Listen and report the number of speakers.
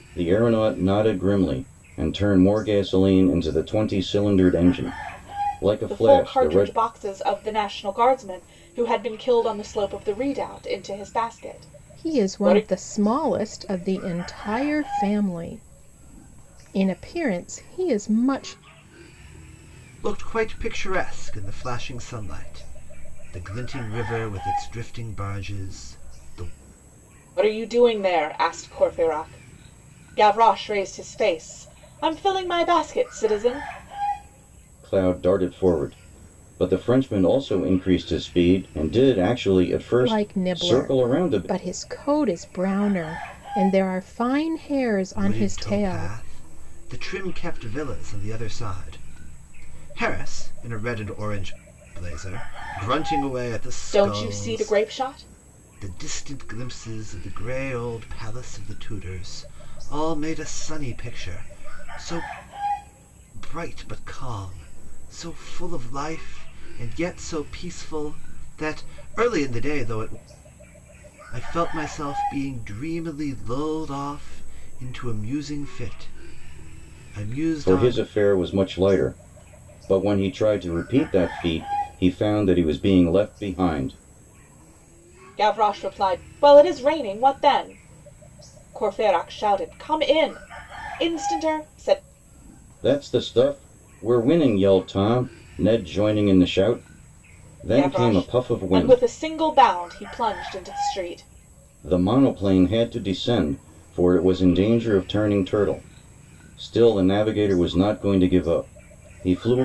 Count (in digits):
4